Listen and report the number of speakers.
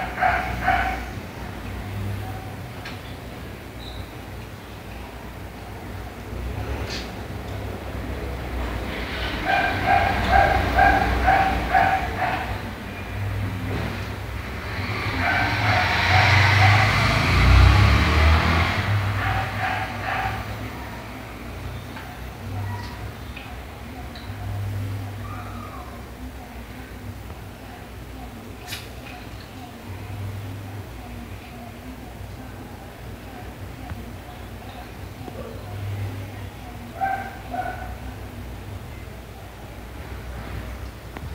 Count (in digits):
0